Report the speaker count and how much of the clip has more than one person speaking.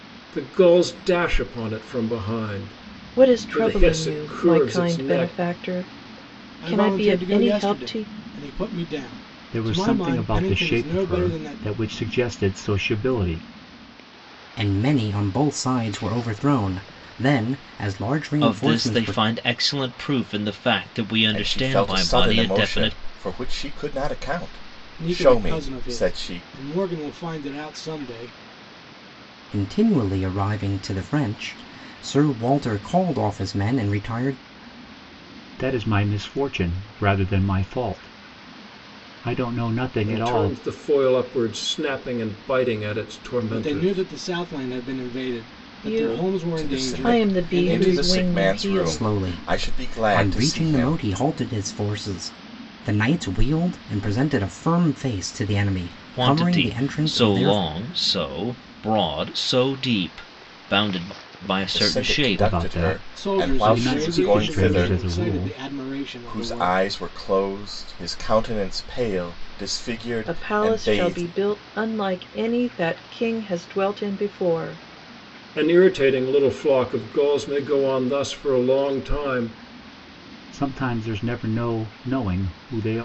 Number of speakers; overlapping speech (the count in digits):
7, about 29%